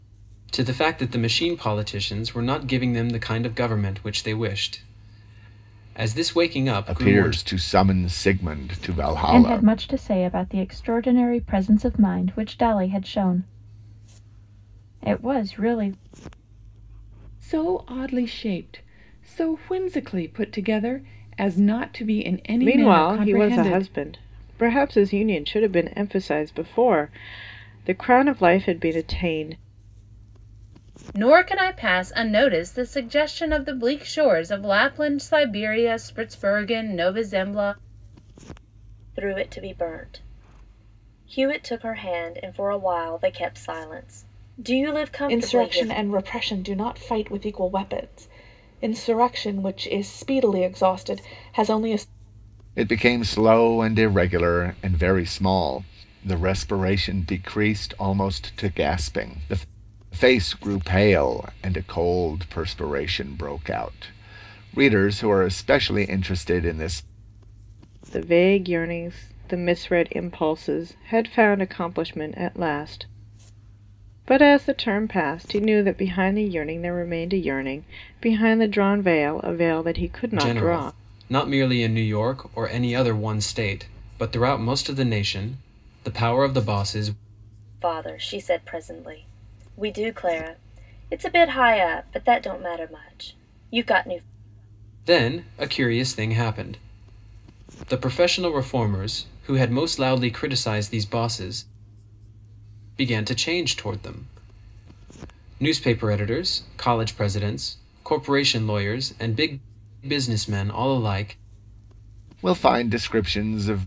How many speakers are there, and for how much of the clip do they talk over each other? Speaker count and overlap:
8, about 3%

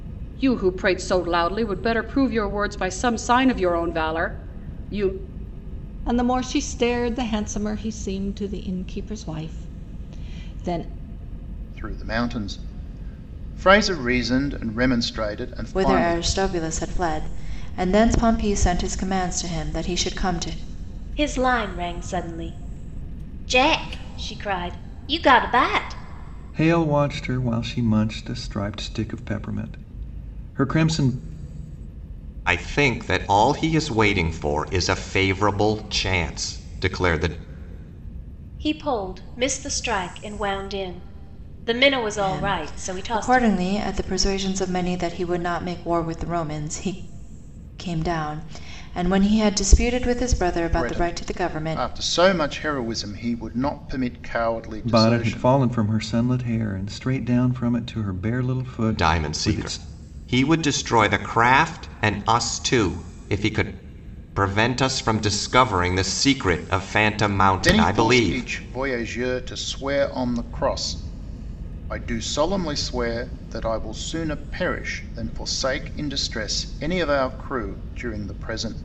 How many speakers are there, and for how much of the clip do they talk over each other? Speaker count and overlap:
7, about 7%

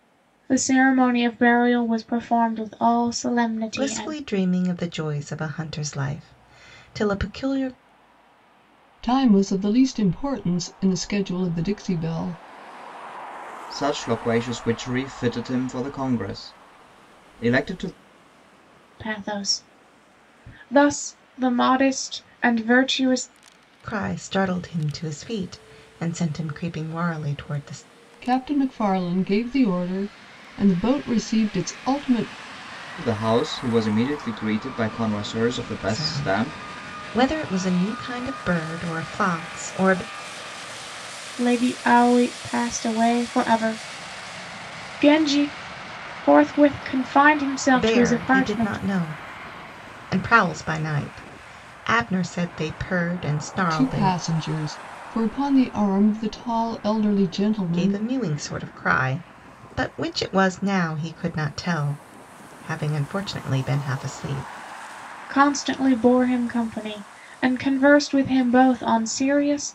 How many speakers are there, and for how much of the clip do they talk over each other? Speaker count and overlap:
4, about 5%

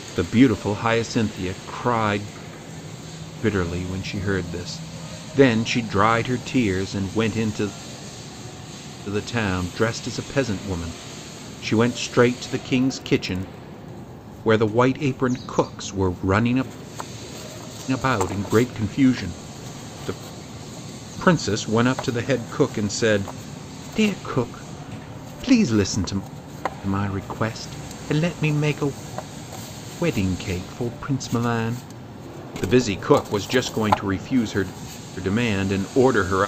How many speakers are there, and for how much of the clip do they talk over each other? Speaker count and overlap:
1, no overlap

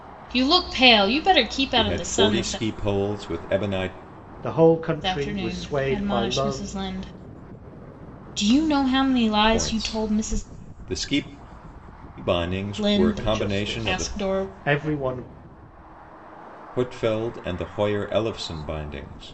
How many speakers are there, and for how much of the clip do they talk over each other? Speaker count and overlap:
3, about 28%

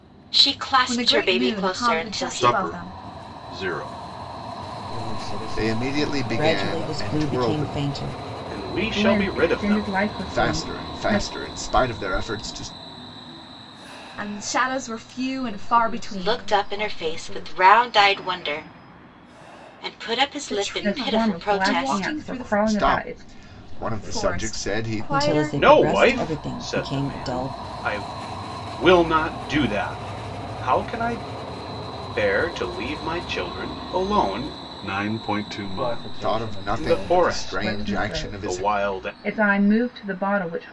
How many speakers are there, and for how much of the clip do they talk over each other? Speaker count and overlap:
8, about 47%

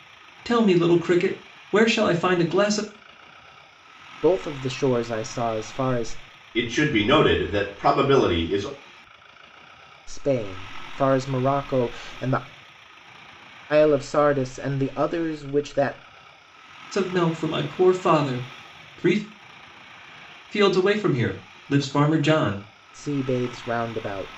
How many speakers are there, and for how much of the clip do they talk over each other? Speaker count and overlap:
3, no overlap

